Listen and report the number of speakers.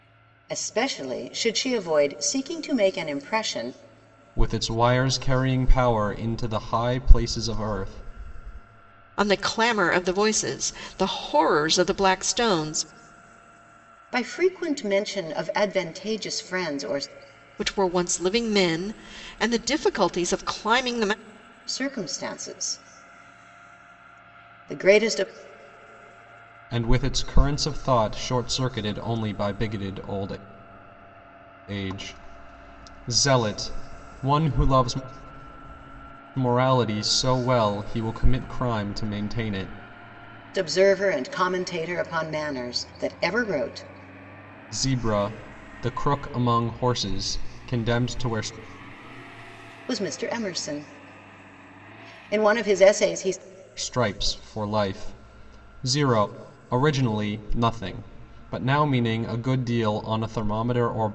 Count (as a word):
three